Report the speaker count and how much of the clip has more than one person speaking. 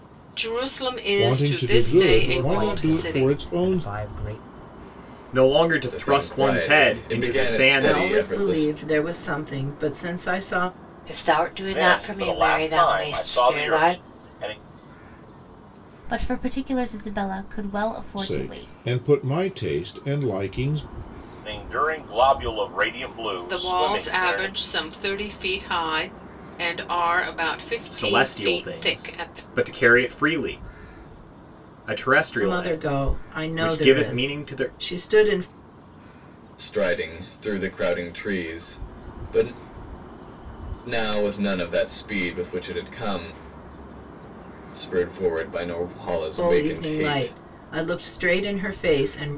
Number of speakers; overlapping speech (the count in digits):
9, about 30%